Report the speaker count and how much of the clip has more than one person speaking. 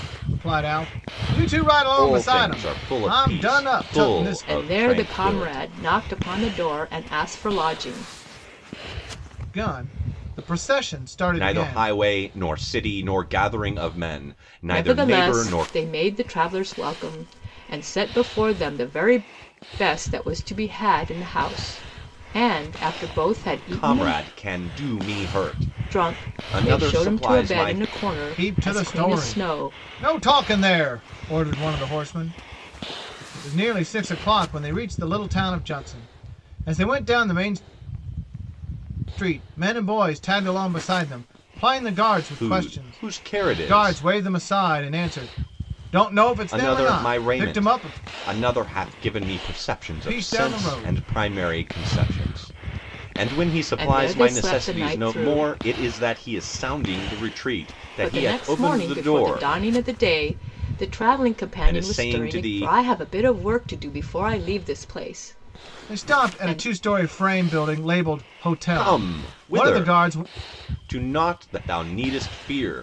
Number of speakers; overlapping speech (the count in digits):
3, about 28%